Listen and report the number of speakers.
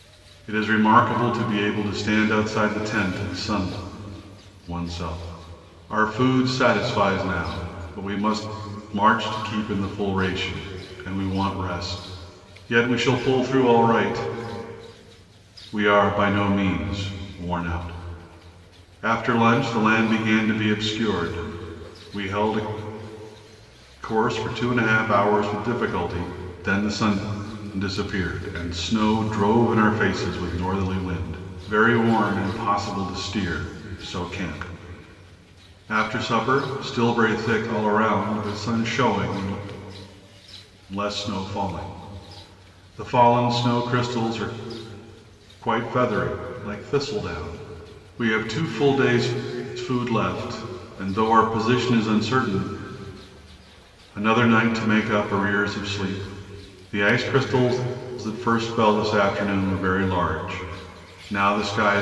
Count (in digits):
1